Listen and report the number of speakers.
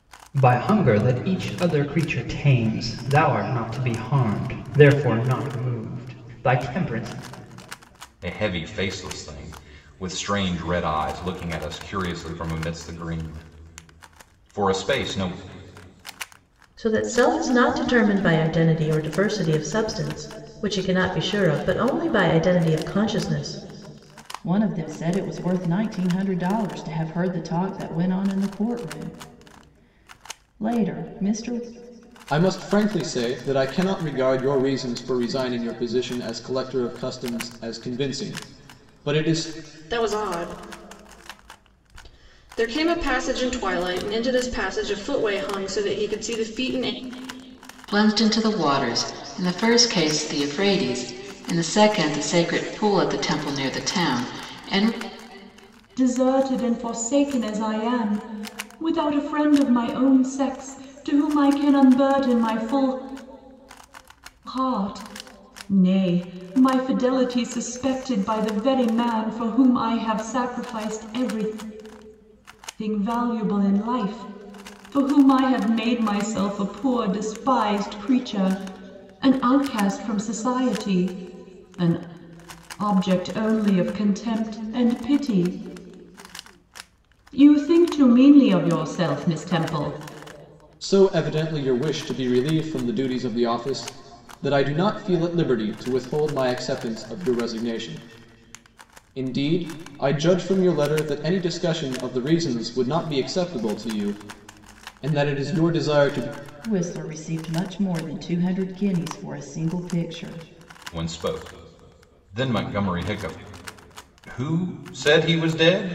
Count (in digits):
8